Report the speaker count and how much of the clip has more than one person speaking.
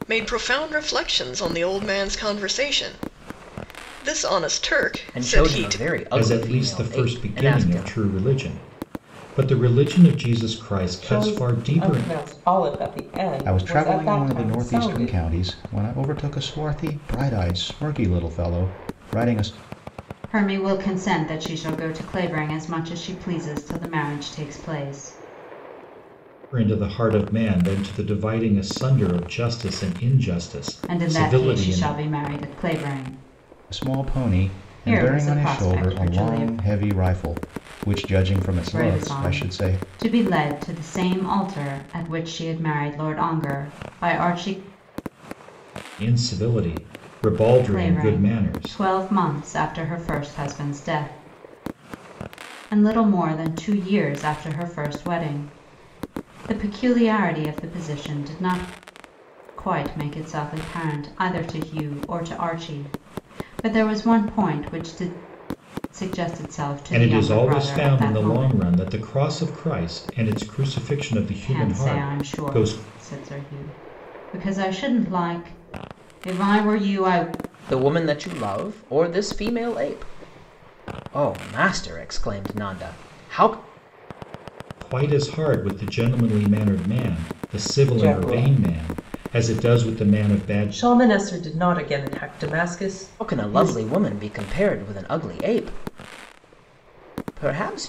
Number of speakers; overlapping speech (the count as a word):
six, about 19%